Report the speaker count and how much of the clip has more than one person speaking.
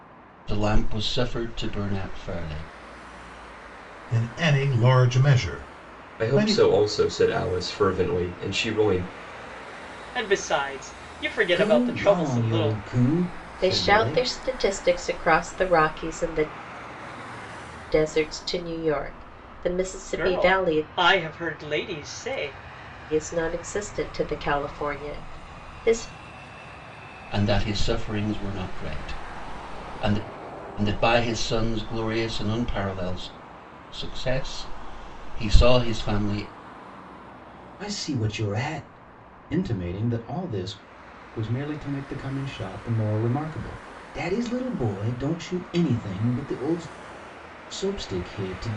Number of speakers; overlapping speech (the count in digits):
6, about 7%